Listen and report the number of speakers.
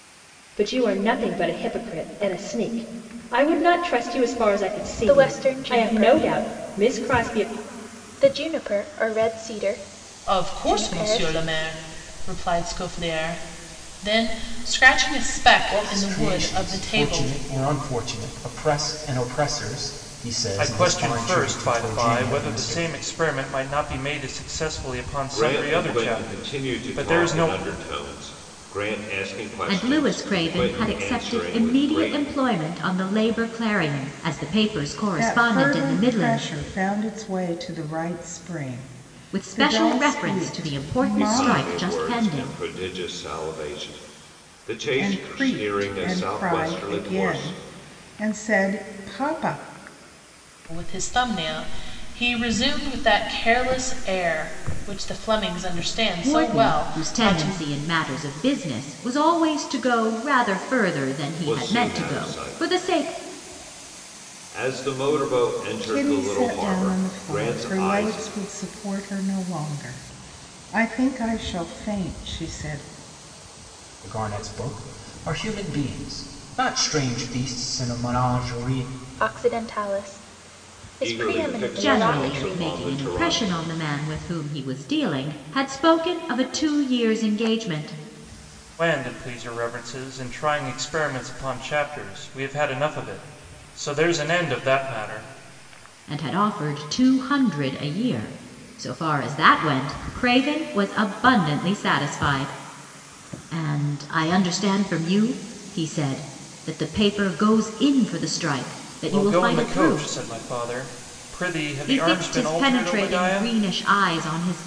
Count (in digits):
8